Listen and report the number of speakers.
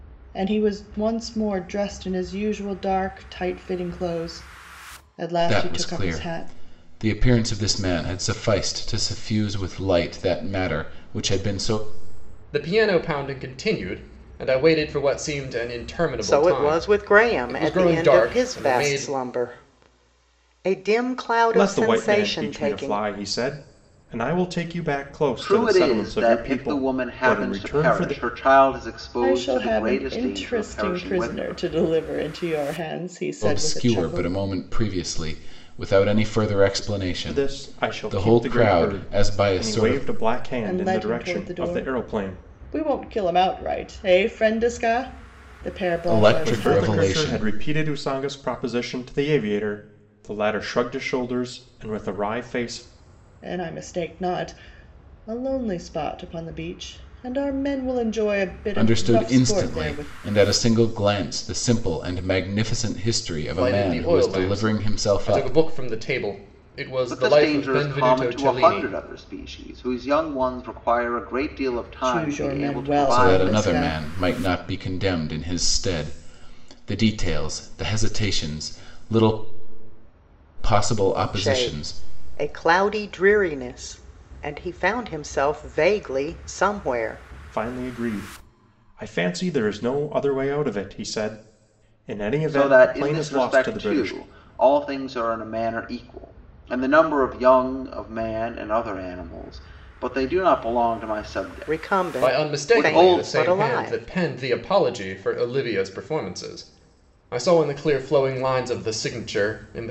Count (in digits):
6